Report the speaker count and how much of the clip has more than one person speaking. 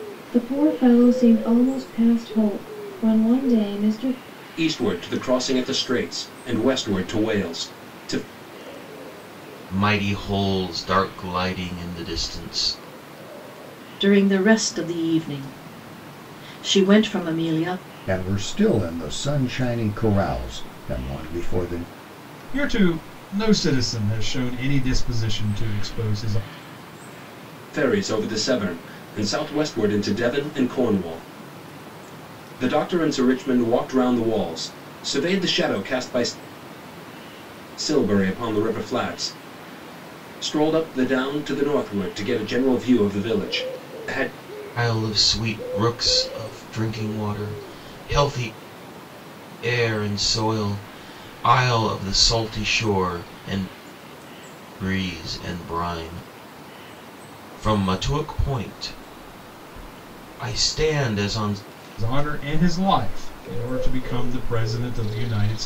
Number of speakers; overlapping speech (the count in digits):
6, no overlap